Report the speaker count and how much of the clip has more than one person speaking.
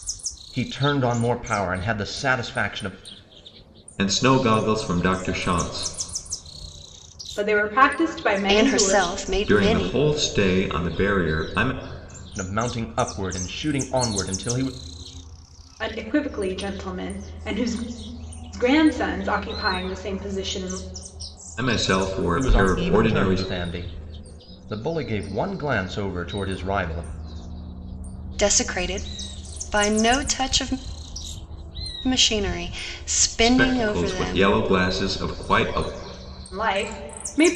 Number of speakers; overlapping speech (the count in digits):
4, about 9%